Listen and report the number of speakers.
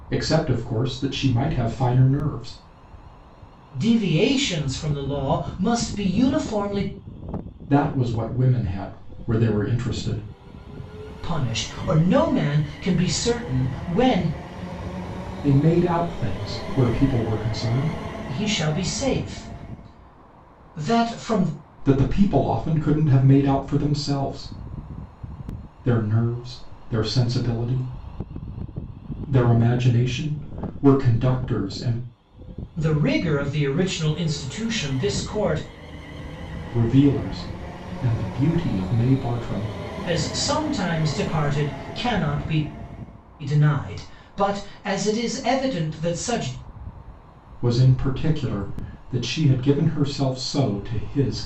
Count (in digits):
2